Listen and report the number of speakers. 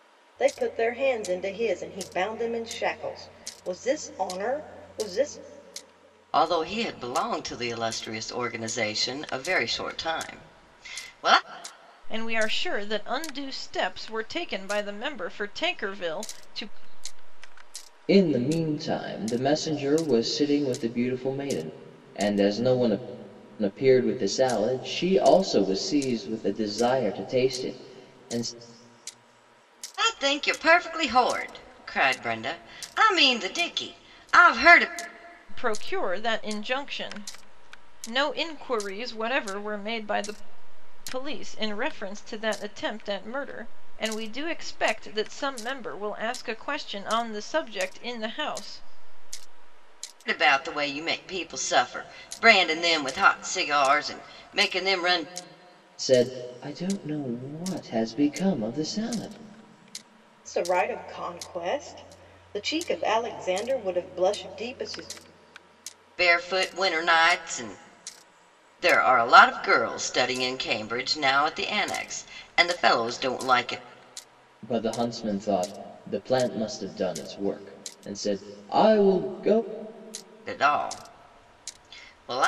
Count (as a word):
four